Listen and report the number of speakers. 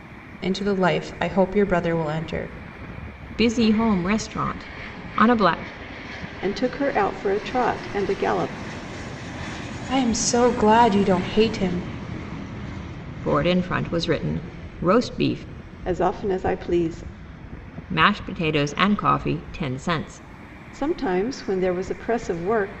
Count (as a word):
three